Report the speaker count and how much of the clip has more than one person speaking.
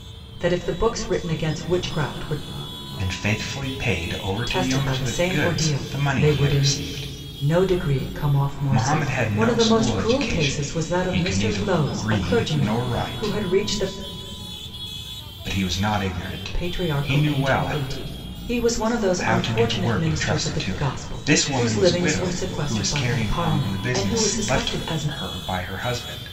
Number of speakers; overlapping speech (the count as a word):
two, about 53%